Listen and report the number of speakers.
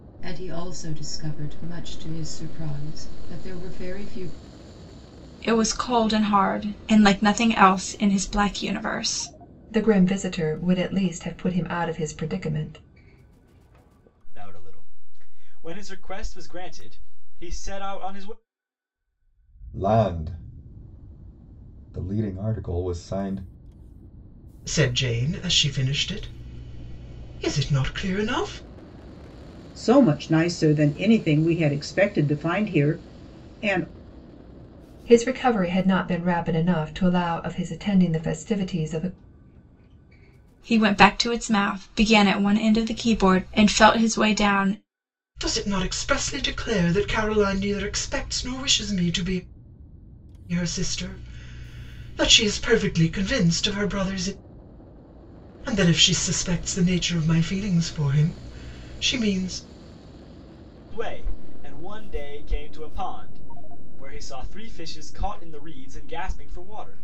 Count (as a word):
seven